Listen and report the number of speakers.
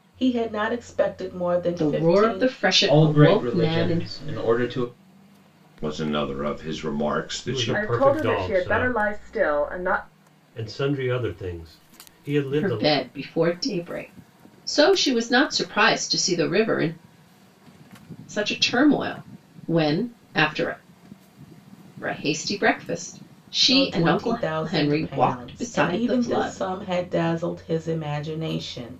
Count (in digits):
6